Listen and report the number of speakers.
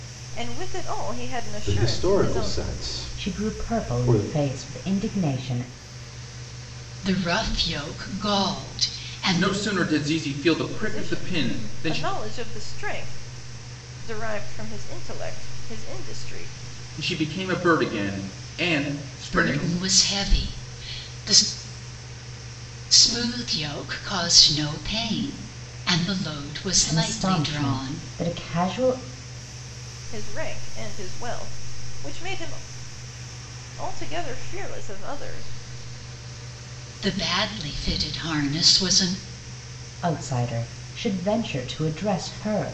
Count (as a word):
five